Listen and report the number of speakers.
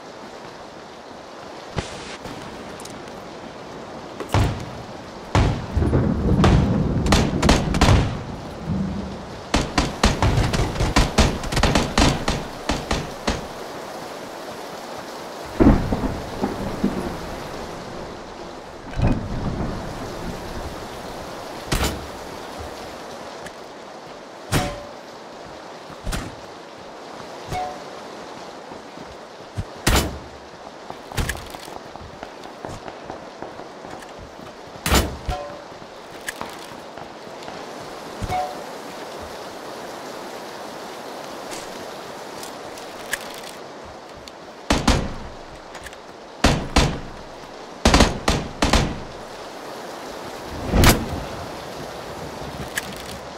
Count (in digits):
0